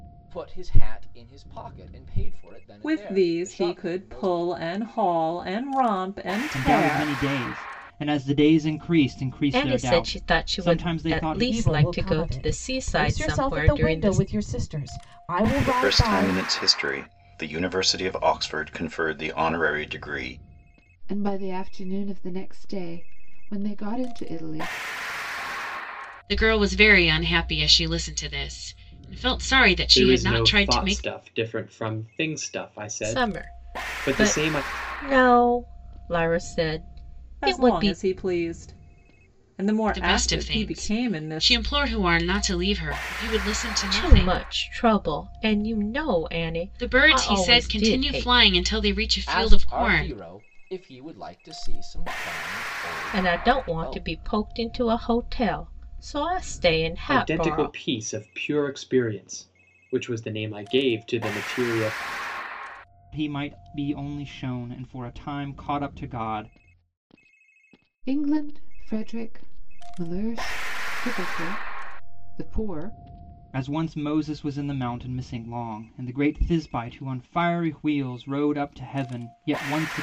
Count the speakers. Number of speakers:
9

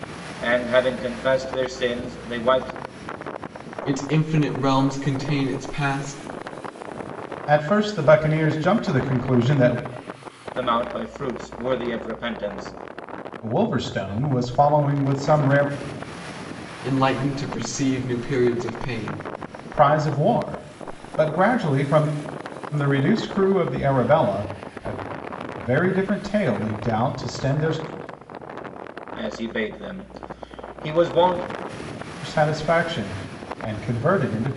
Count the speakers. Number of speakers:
3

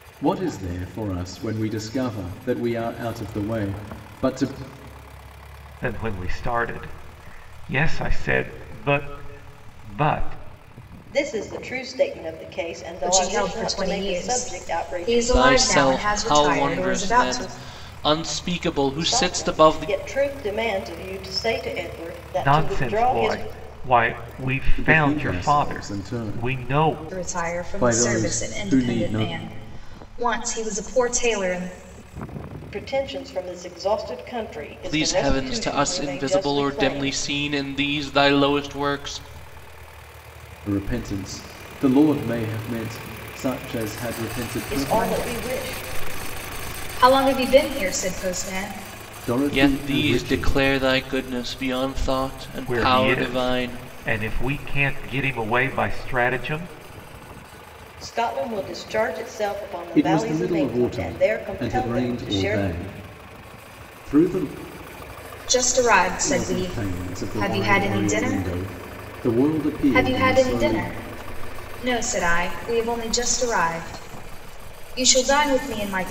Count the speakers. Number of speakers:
5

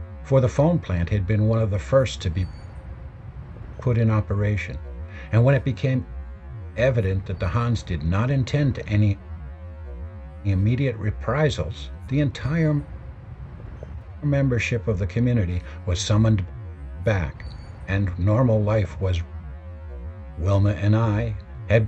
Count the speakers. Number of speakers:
1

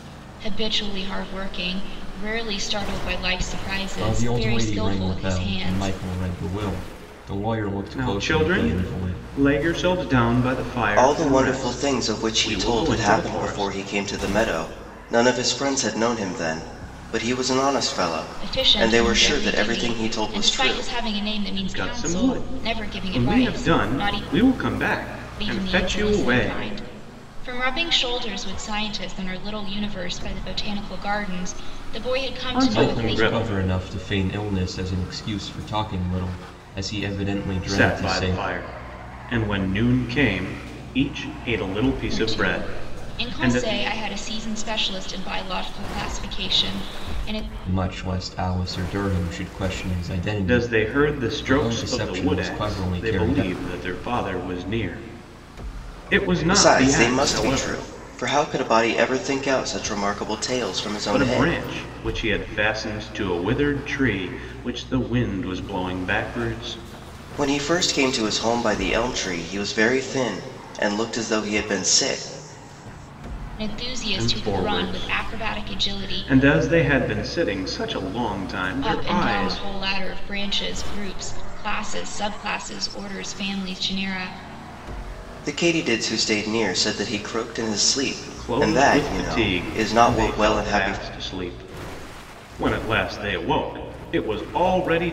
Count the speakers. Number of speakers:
4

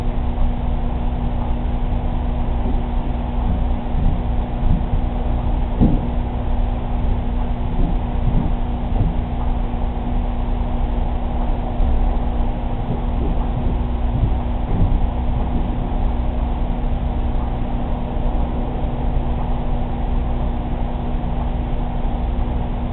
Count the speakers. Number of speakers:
0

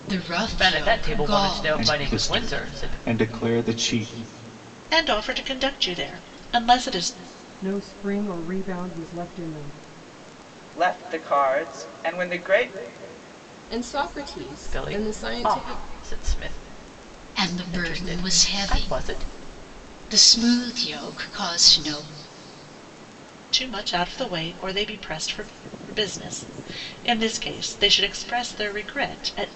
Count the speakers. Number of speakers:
7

